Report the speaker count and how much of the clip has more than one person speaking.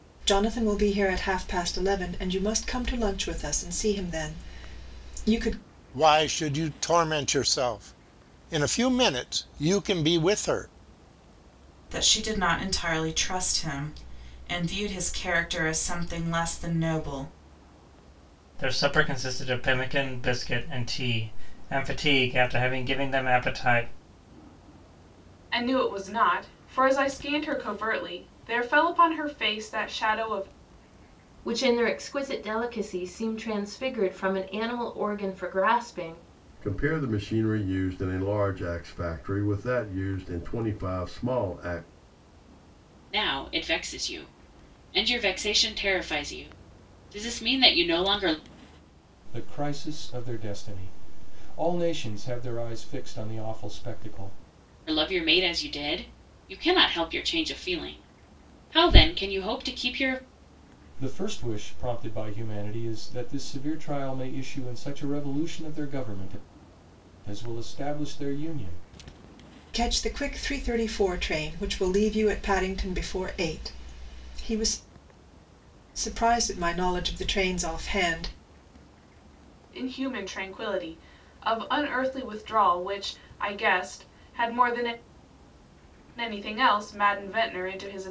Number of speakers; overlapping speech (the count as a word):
nine, no overlap